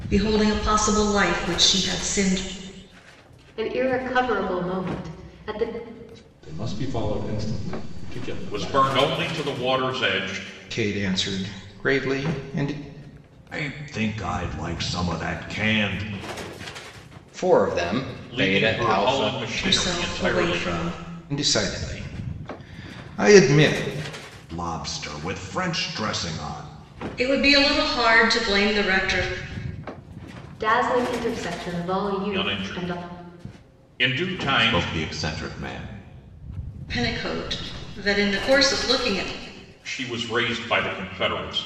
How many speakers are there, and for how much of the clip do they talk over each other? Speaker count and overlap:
7, about 9%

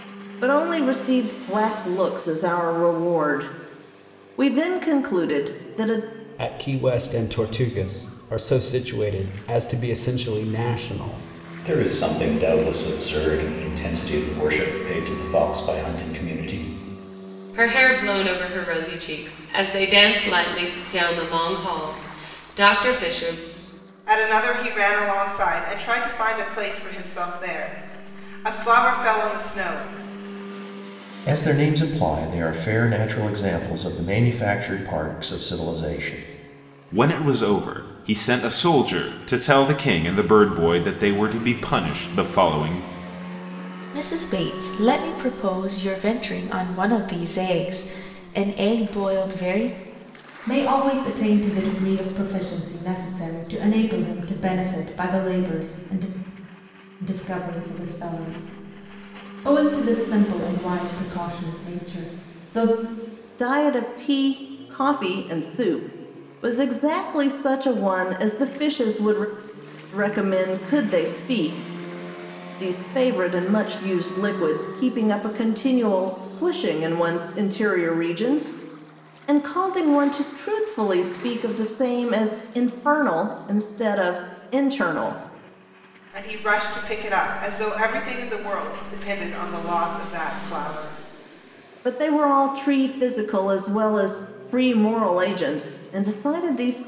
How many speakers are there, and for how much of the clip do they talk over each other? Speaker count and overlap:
9, no overlap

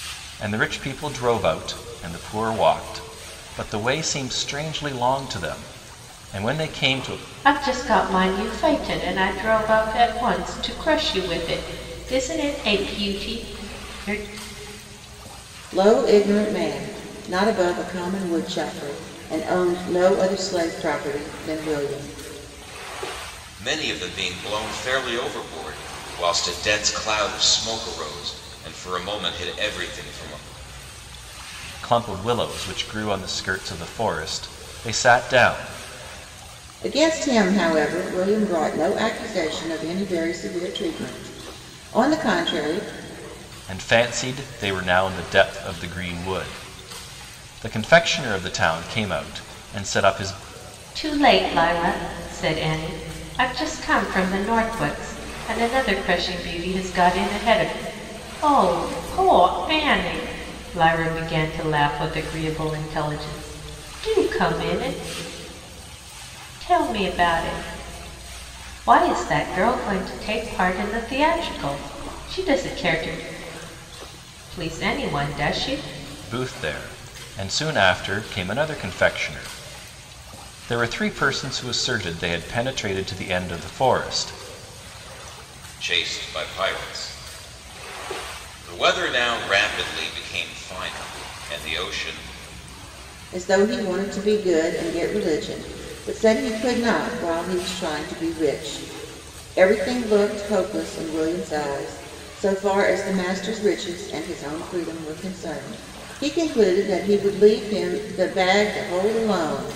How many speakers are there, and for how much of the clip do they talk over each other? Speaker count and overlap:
4, no overlap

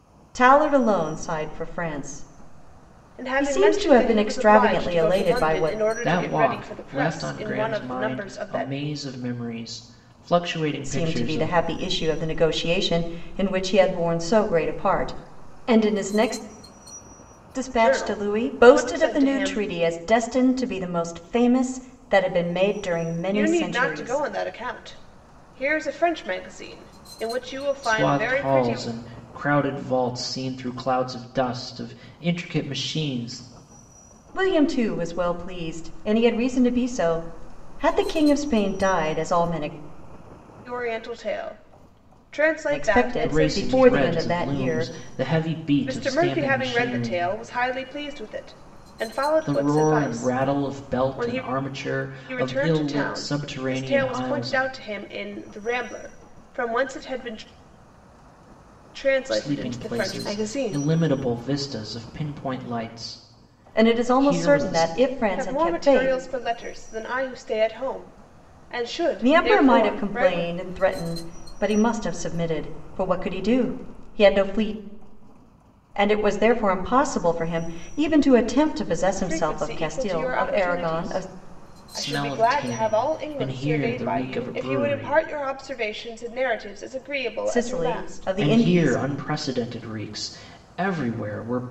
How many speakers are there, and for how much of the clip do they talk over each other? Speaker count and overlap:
3, about 33%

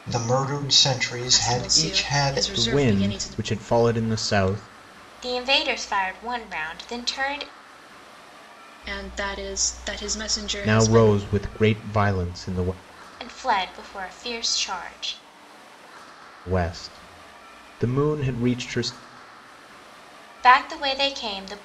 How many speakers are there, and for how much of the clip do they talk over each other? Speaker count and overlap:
4, about 12%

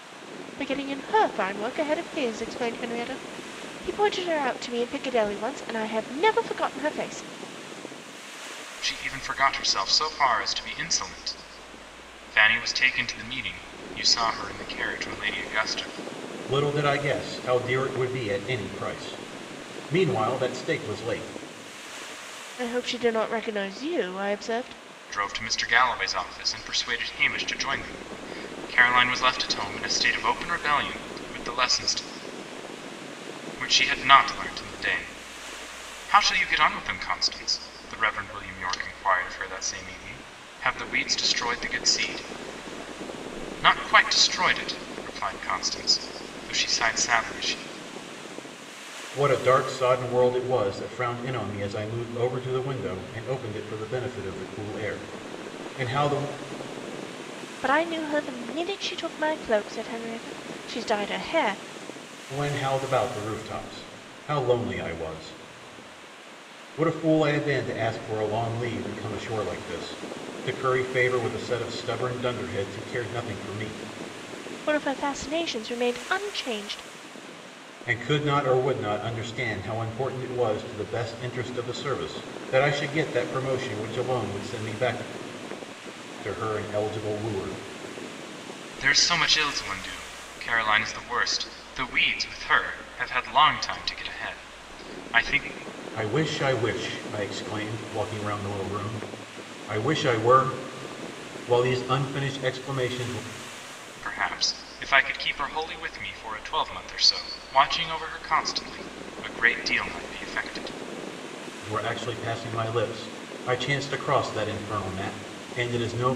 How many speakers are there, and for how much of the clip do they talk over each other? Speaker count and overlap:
3, no overlap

